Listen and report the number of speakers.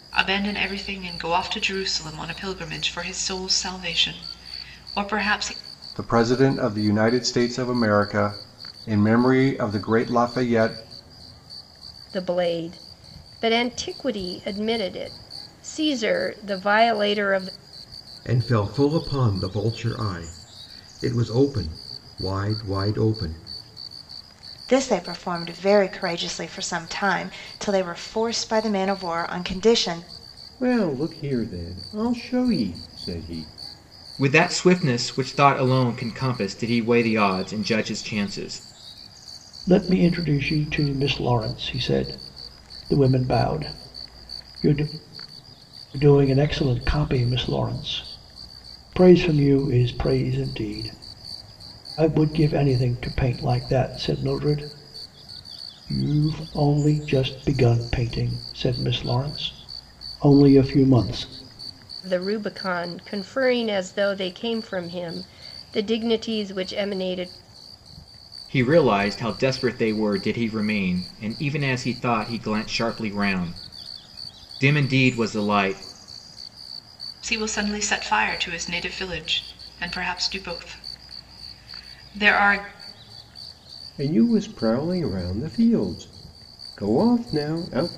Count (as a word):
eight